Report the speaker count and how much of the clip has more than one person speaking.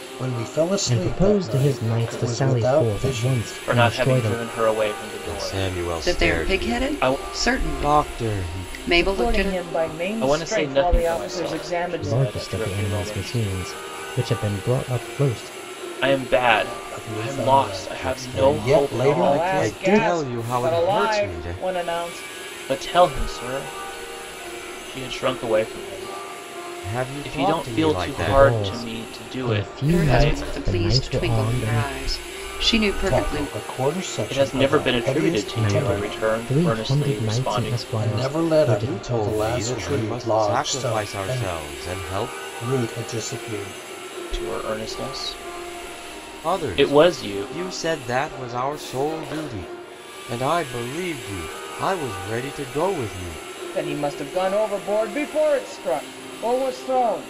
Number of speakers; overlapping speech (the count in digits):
6, about 51%